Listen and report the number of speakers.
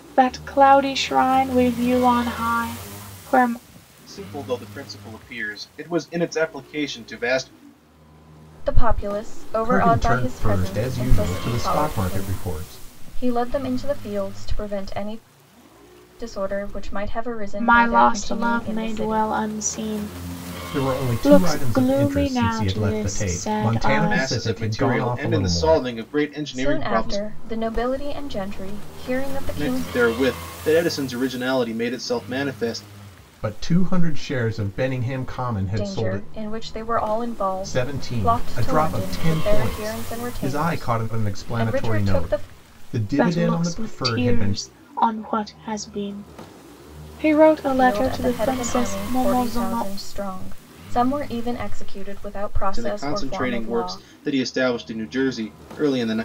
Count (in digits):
4